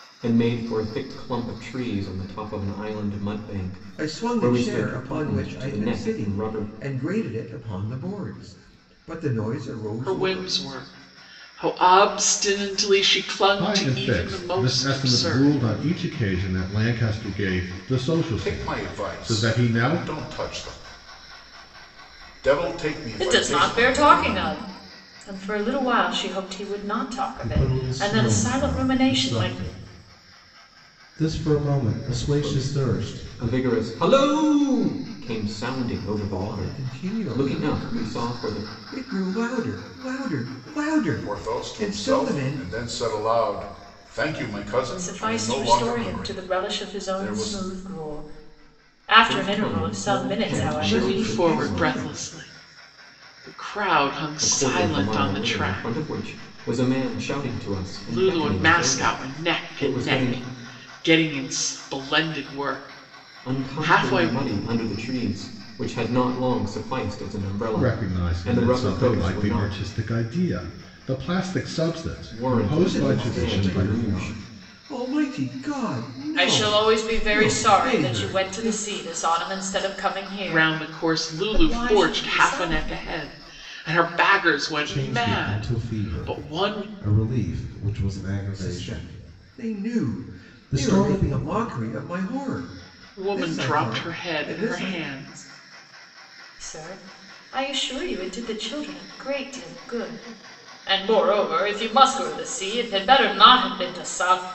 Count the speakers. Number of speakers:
7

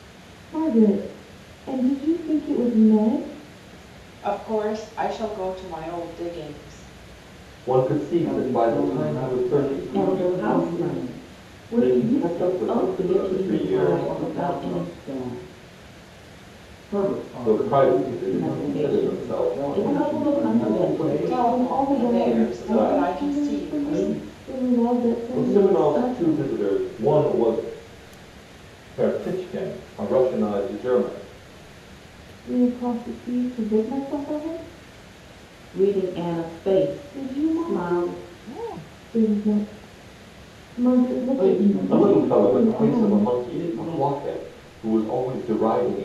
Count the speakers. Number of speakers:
5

